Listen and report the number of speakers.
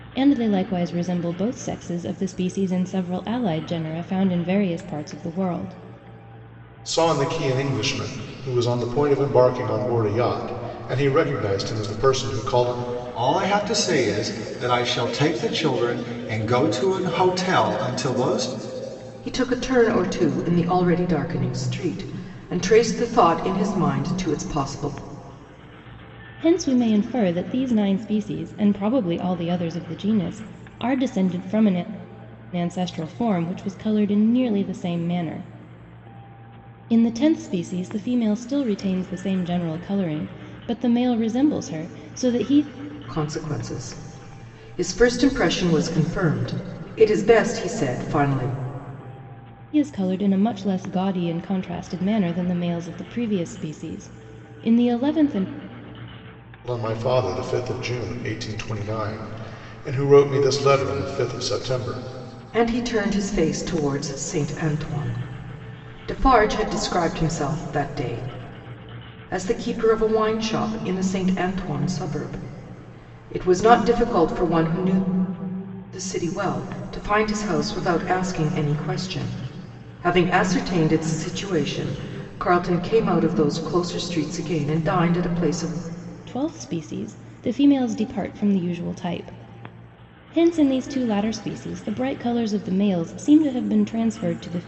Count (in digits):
4